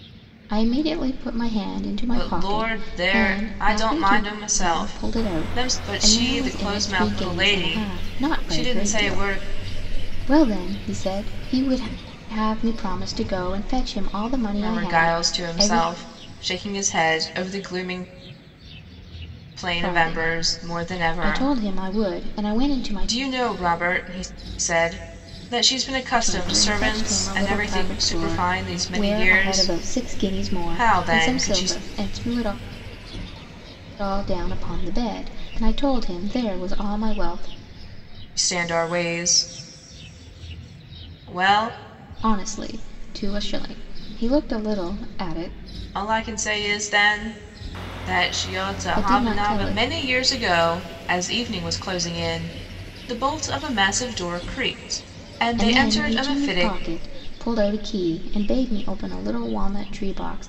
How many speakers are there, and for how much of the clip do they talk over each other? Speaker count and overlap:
two, about 32%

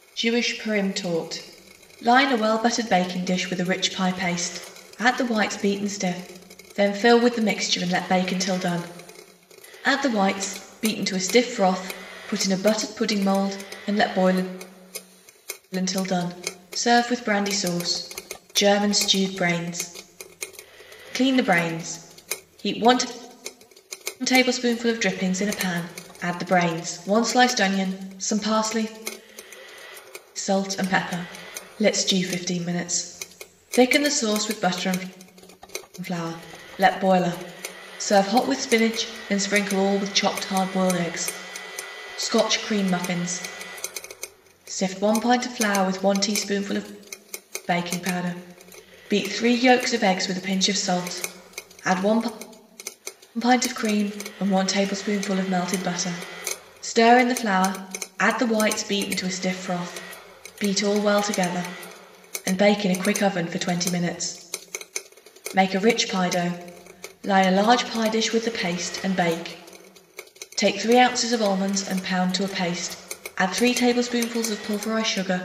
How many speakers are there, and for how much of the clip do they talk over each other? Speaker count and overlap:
one, no overlap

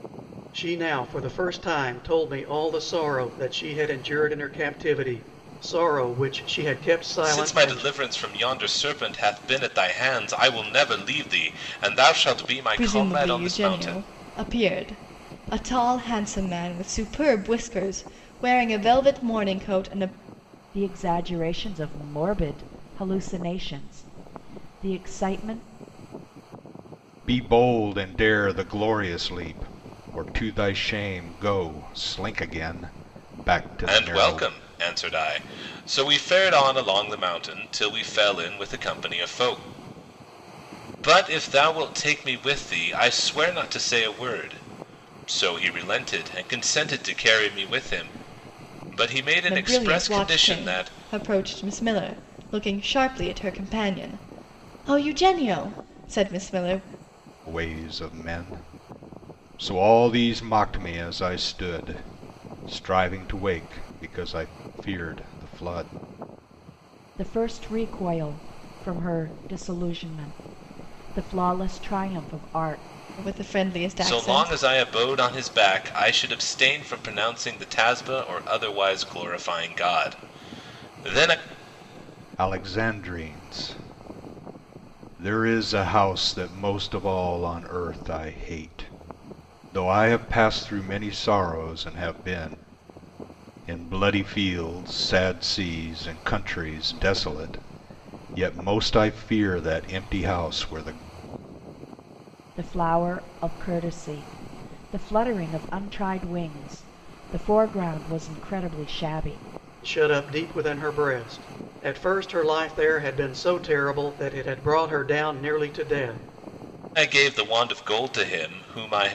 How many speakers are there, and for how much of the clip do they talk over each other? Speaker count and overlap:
five, about 4%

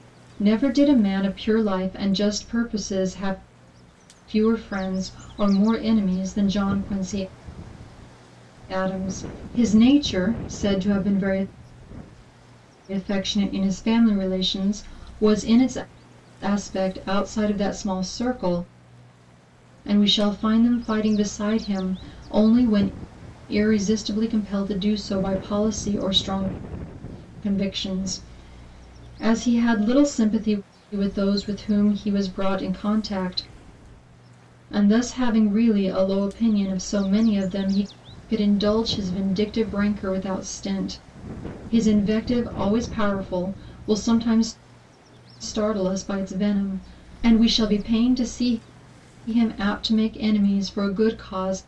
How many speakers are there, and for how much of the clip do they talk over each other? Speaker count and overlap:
one, no overlap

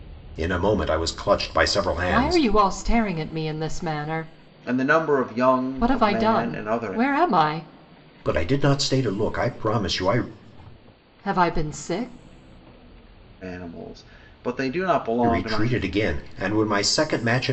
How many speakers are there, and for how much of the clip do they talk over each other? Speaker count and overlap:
three, about 13%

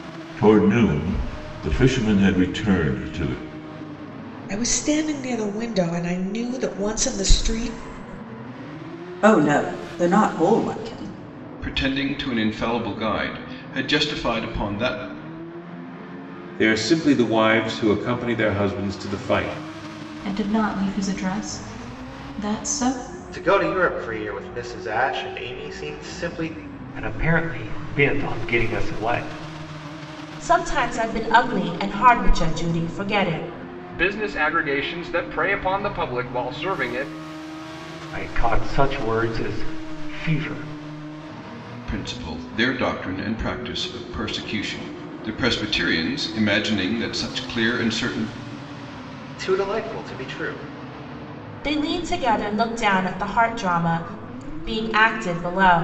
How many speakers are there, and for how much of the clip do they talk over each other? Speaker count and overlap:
ten, no overlap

